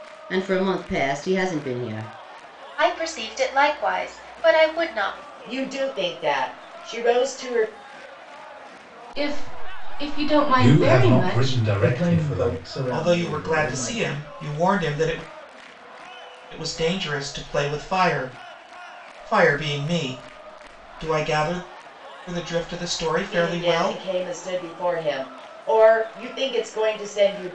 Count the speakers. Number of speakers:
7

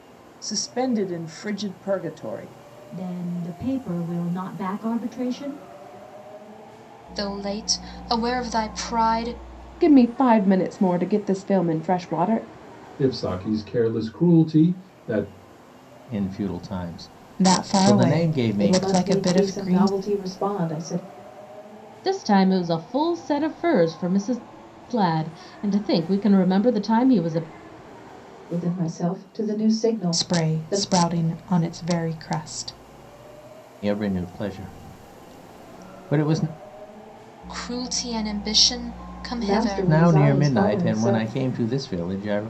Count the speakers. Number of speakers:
9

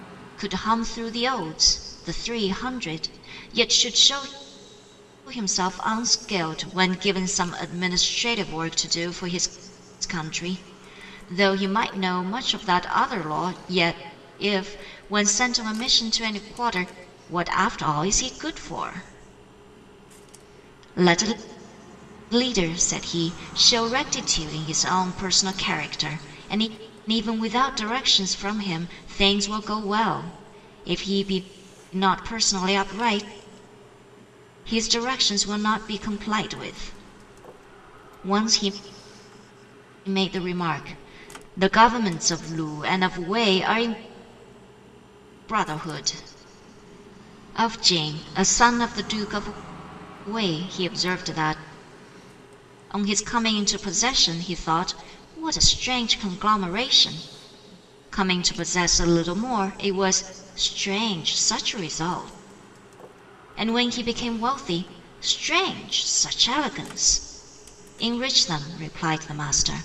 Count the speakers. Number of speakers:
1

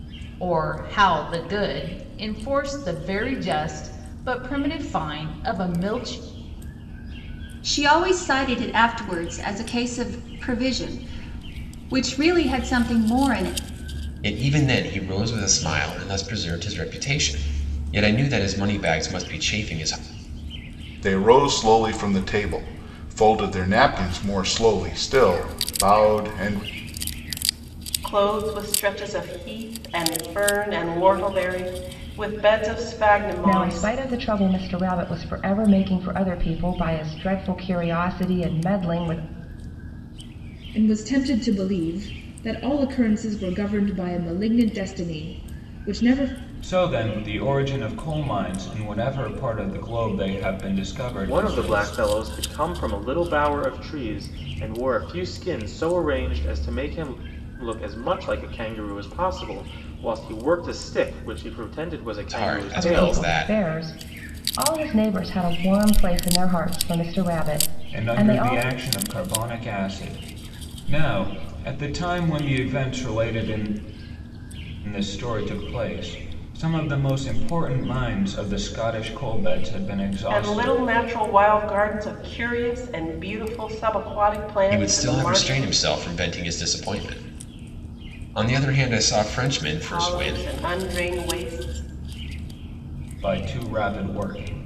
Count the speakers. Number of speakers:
9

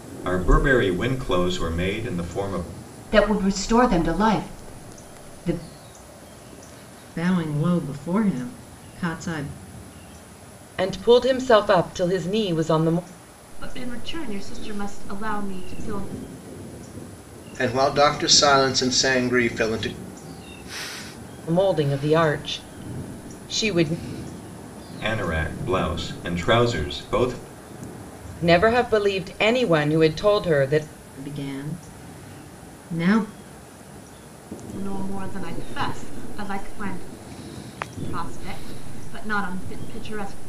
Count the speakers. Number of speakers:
6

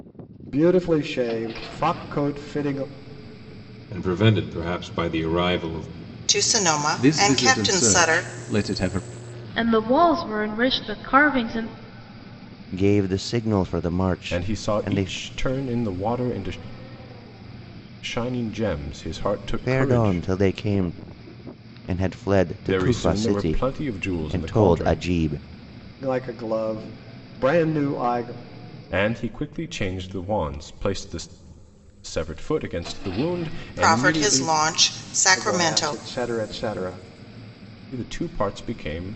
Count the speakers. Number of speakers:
7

